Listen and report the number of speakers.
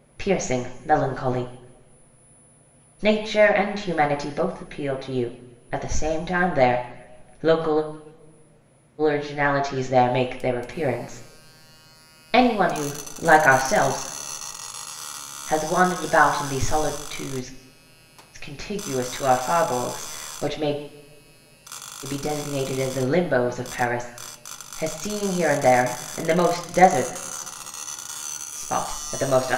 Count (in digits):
1